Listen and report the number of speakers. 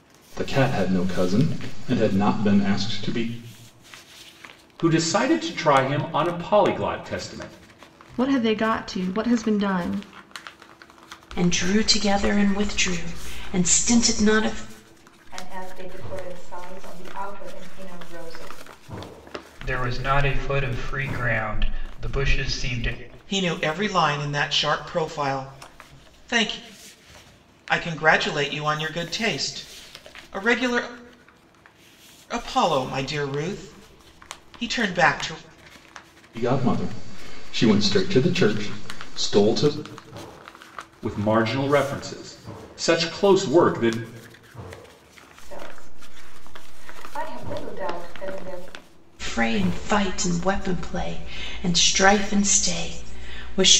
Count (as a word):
seven